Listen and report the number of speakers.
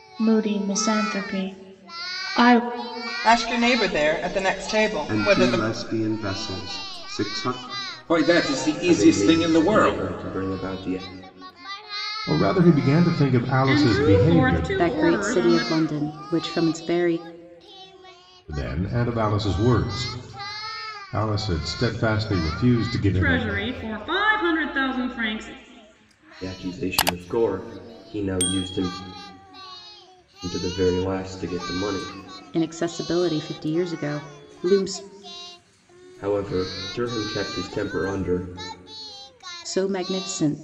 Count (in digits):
8